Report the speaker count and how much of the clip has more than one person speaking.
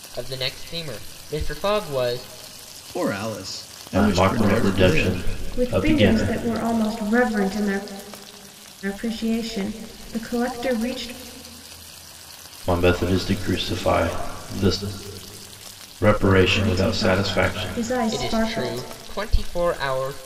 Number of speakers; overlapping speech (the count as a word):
four, about 22%